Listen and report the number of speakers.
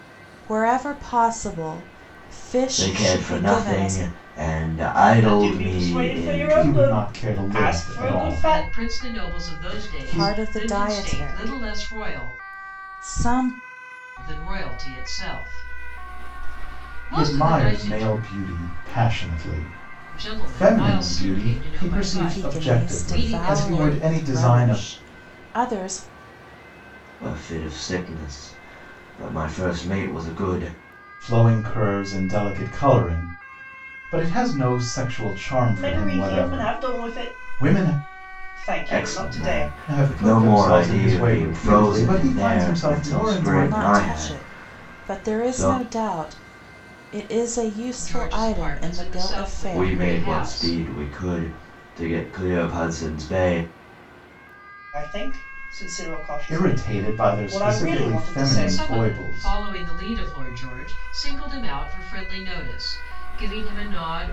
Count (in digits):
5